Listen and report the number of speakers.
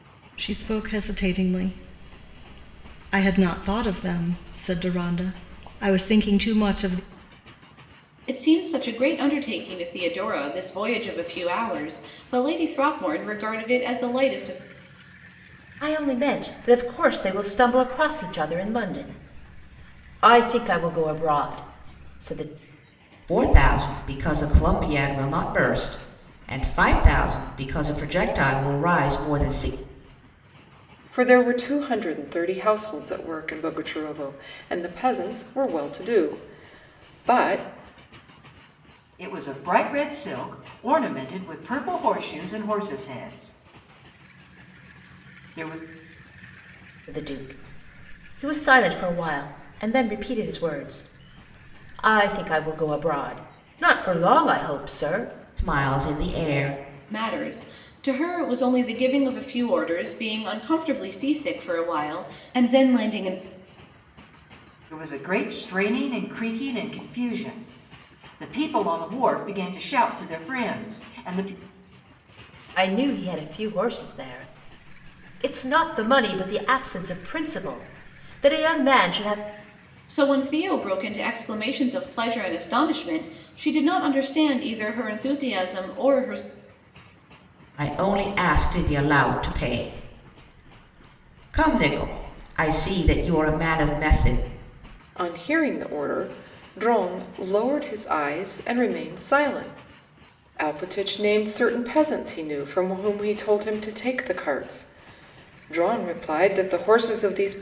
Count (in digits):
6